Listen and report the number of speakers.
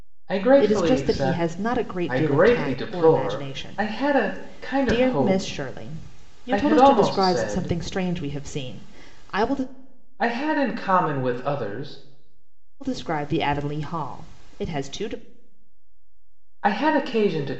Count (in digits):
2